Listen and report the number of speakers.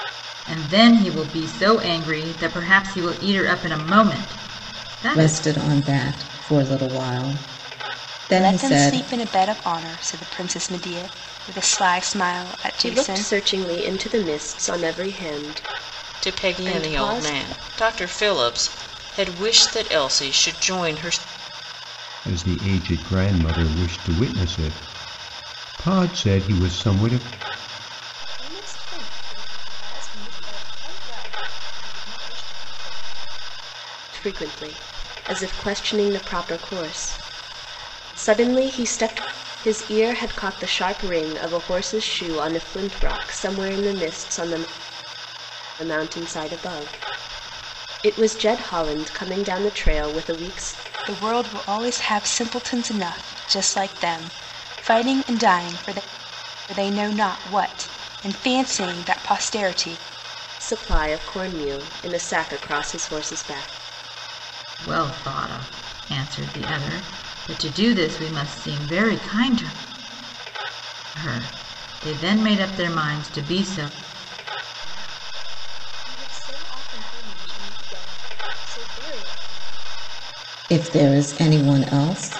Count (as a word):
seven